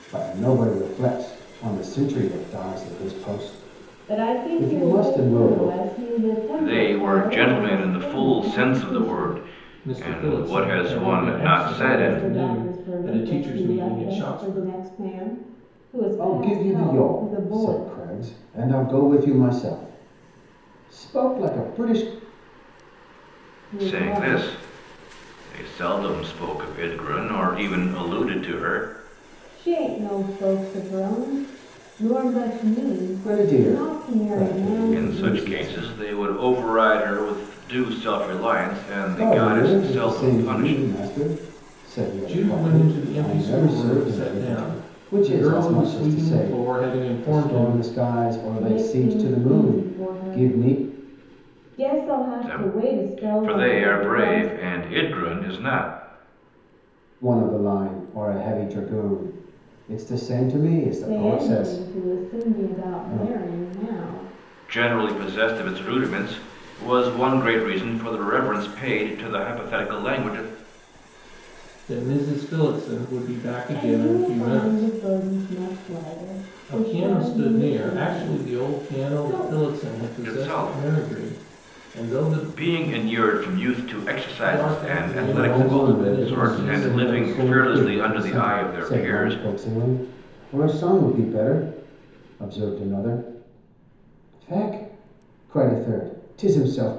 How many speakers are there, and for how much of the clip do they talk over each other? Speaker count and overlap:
4, about 41%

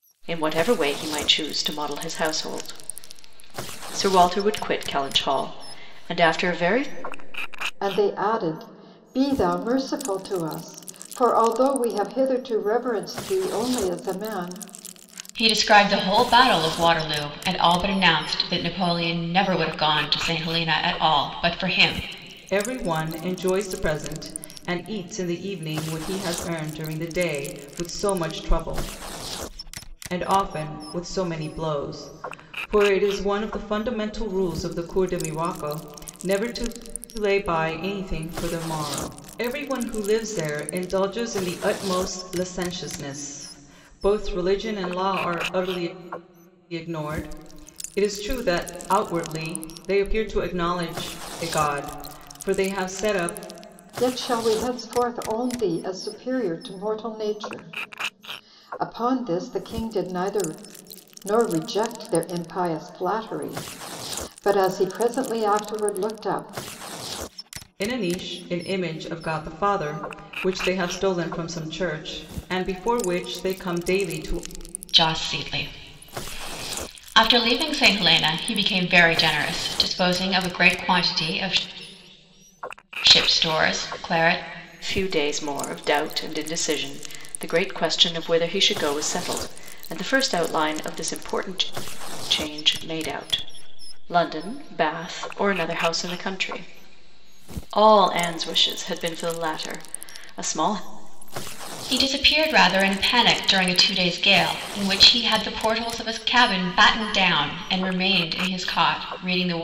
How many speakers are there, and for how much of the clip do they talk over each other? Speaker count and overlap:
4, no overlap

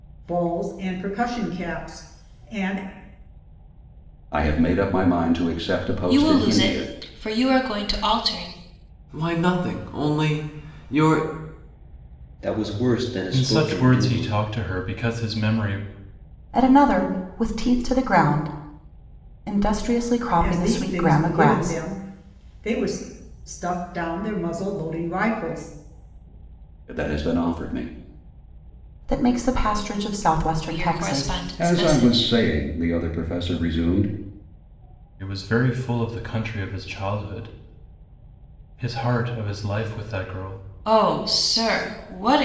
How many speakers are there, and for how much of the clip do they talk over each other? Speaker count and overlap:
7, about 11%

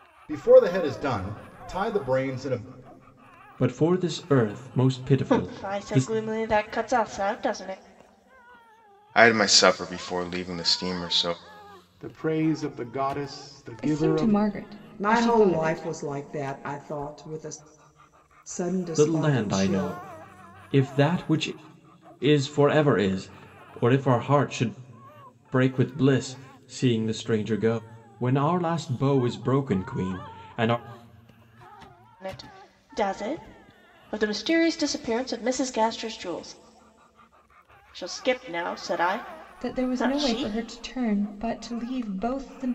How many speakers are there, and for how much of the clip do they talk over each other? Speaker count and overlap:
7, about 11%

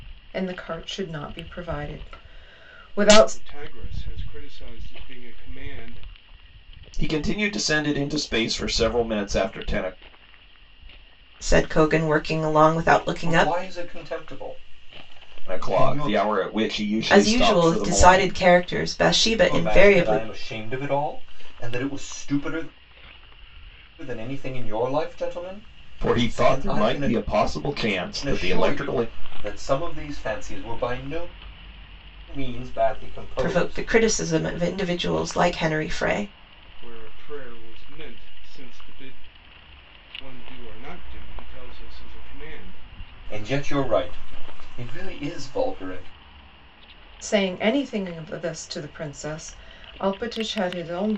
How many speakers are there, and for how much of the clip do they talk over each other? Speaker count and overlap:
5, about 12%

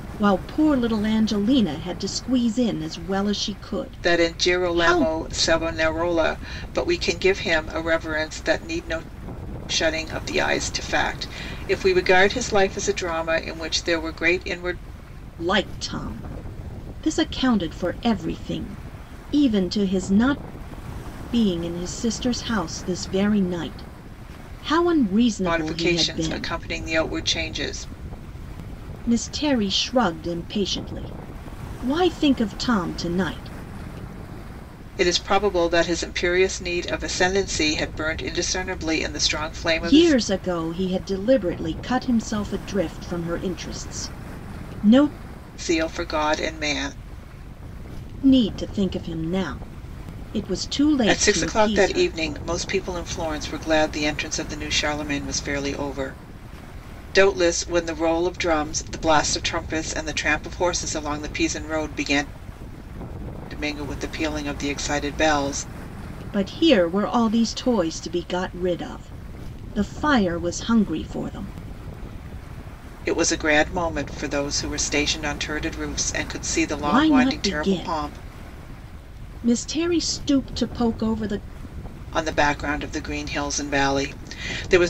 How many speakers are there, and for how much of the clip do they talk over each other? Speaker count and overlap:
2, about 6%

